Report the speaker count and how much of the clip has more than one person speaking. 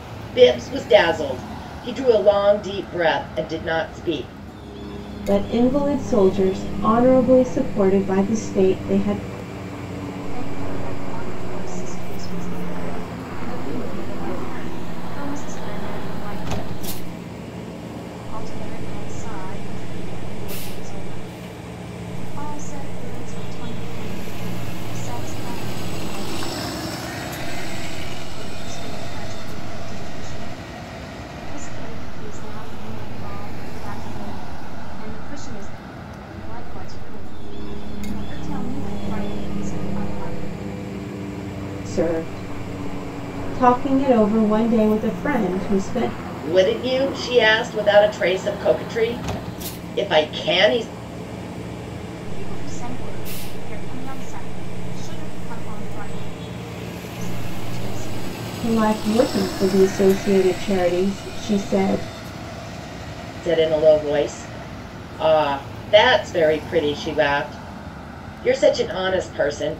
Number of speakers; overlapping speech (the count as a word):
three, no overlap